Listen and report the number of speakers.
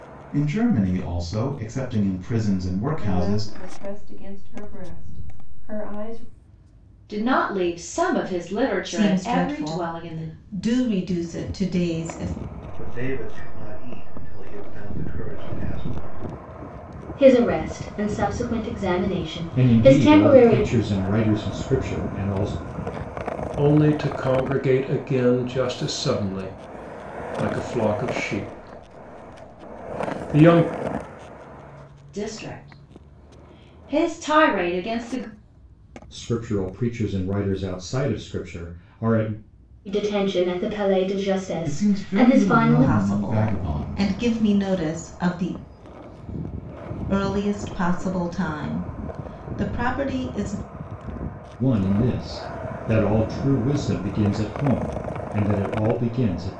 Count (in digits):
8